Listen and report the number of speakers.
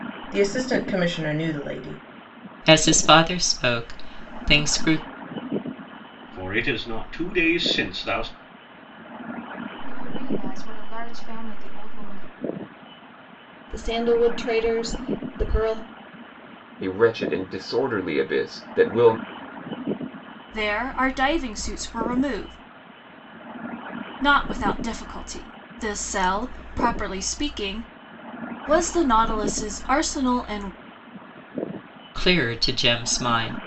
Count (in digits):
7